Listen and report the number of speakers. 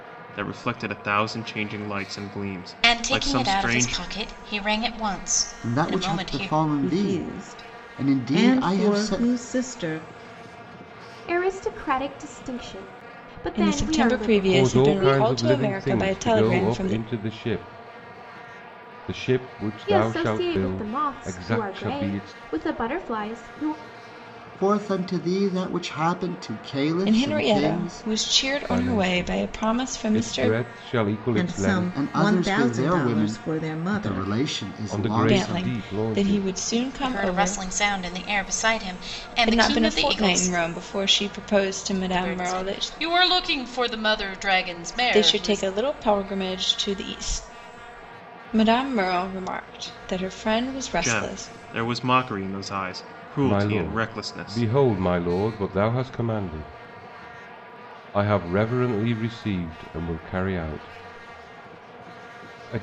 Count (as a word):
seven